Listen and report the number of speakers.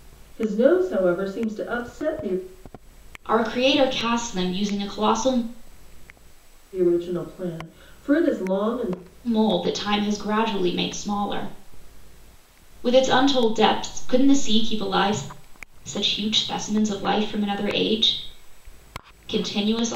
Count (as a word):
two